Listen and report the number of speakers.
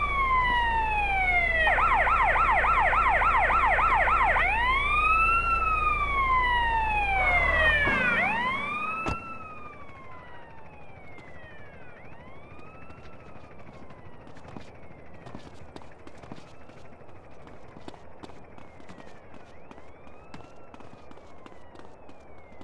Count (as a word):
zero